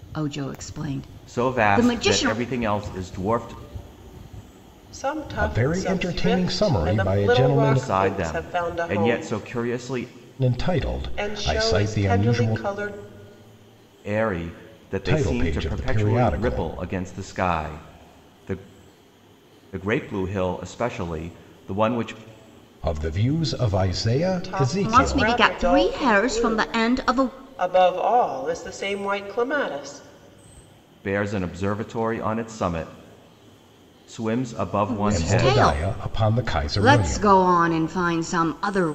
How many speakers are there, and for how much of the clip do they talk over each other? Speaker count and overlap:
4, about 31%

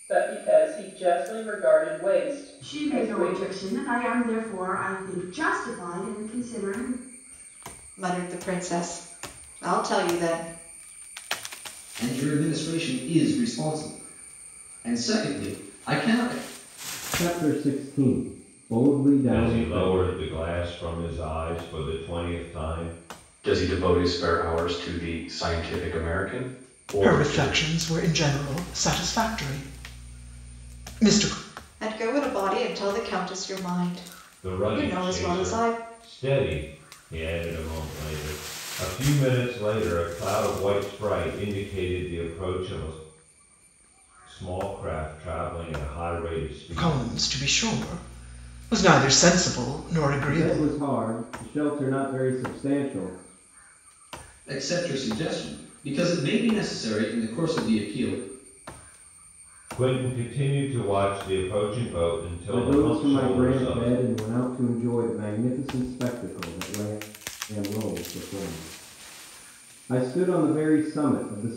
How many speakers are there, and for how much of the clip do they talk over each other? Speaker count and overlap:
8, about 9%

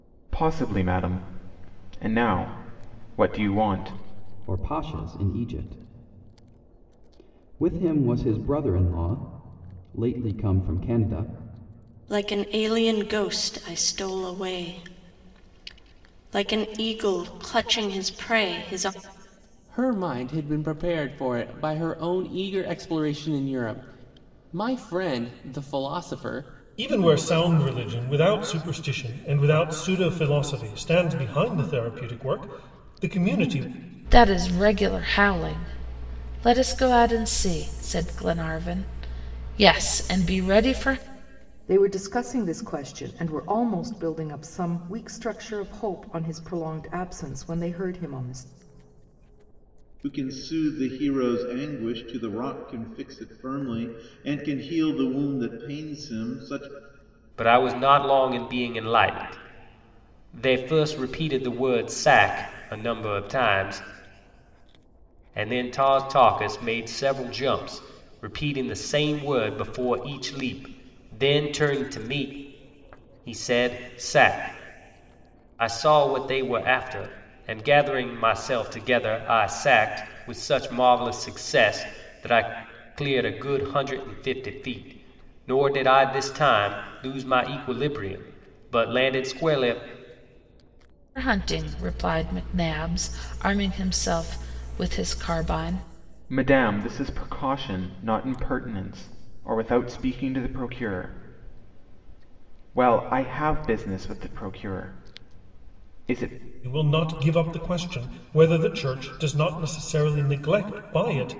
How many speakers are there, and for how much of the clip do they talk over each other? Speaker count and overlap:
9, no overlap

